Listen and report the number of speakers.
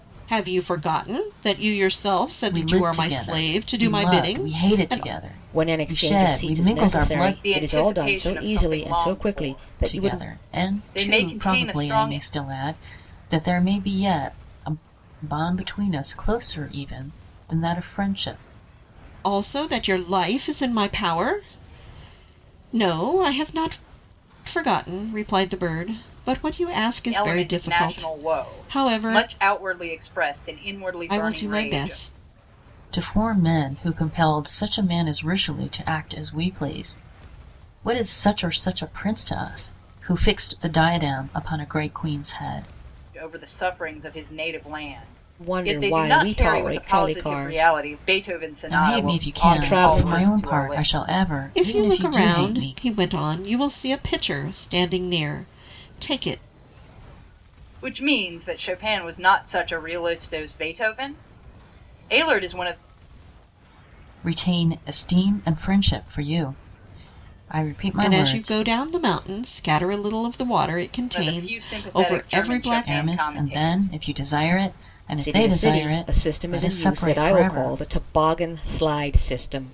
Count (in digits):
4